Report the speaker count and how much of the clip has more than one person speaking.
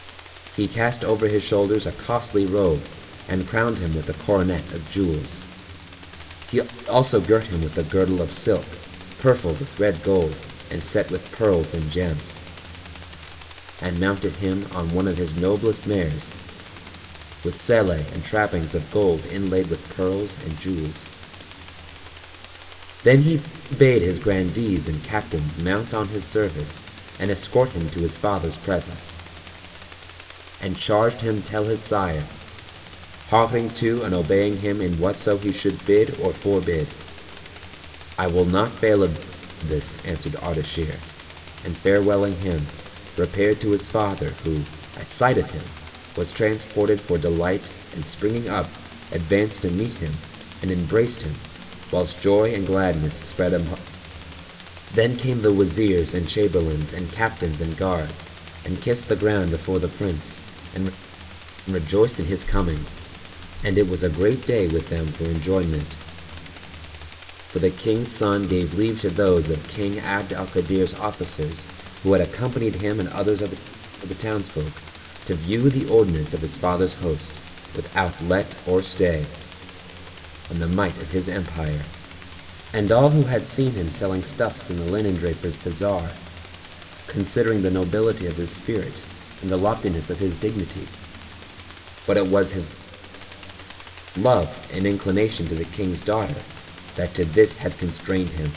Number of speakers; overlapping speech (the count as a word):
one, no overlap